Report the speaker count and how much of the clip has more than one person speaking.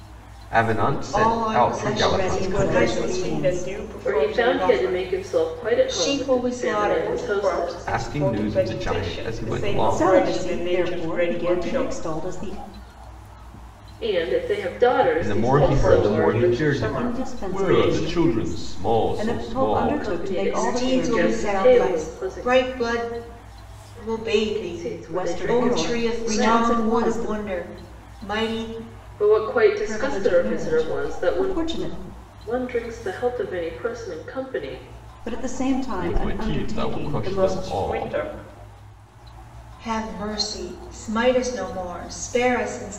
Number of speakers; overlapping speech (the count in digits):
5, about 58%